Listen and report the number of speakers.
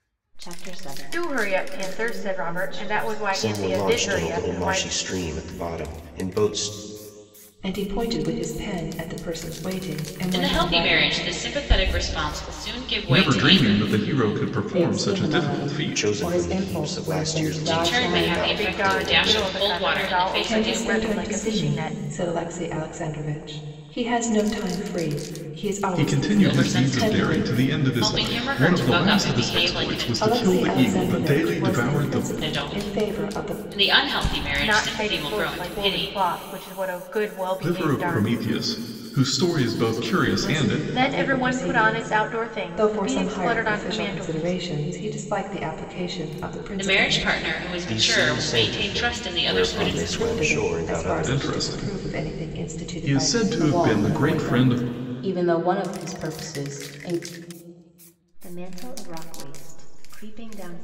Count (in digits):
7